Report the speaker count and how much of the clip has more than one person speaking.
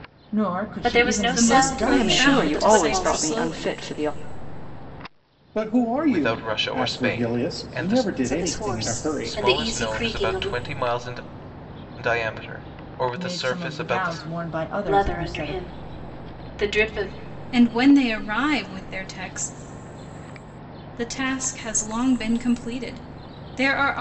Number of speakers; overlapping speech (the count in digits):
6, about 38%